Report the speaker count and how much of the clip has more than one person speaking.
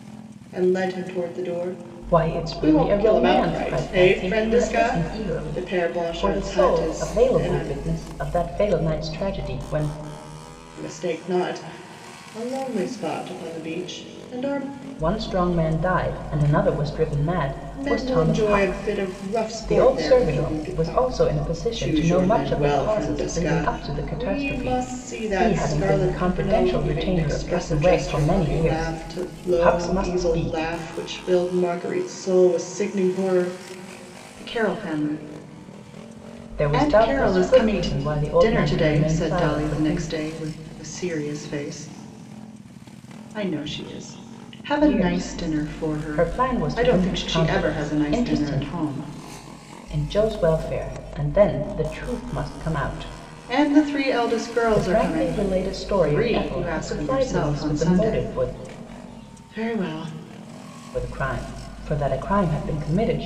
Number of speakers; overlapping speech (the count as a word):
two, about 42%